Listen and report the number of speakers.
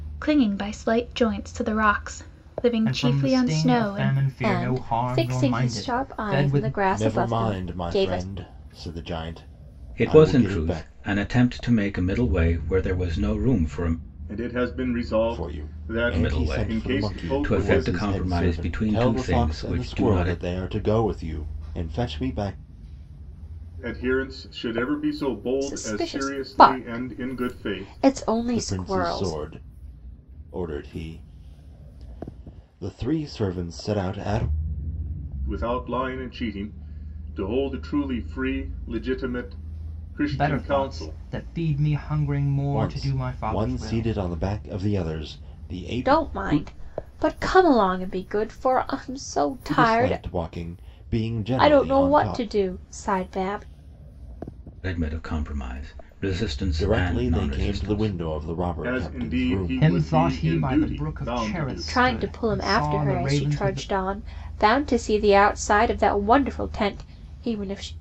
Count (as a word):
six